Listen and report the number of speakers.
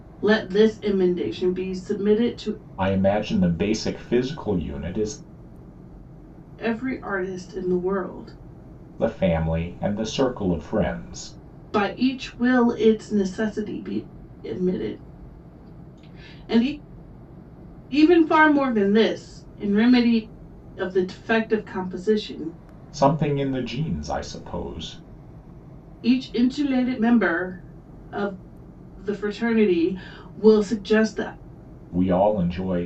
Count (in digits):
2